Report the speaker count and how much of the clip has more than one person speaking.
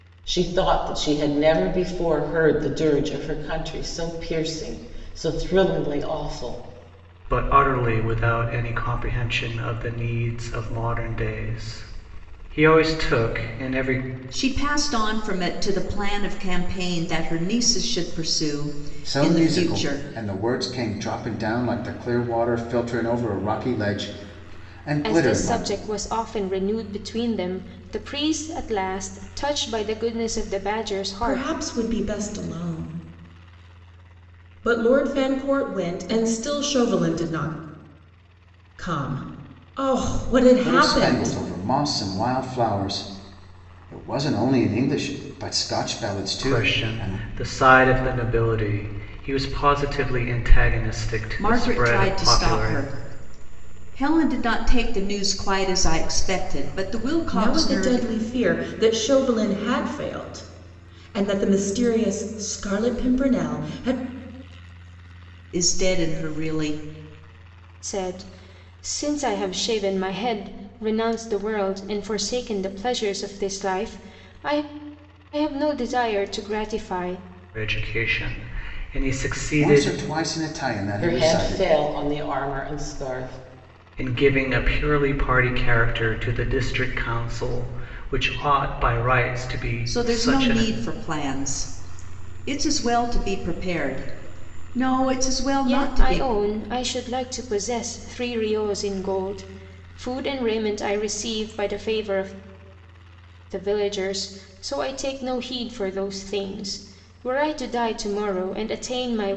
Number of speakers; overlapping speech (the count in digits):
6, about 8%